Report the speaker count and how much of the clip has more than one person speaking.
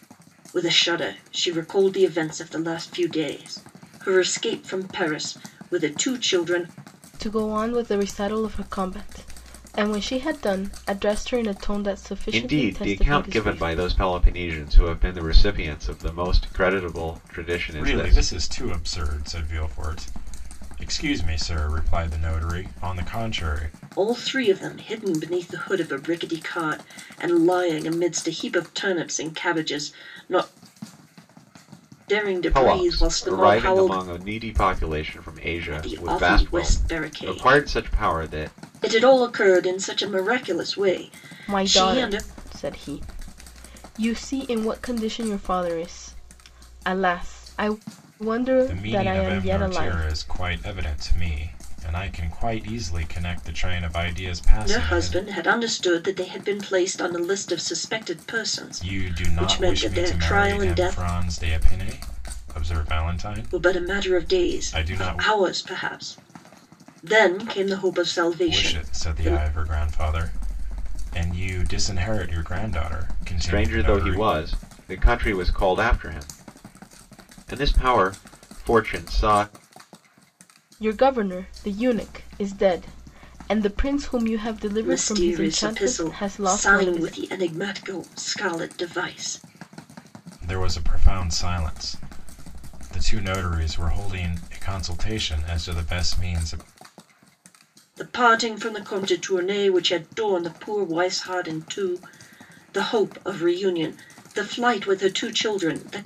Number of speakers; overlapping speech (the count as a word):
four, about 17%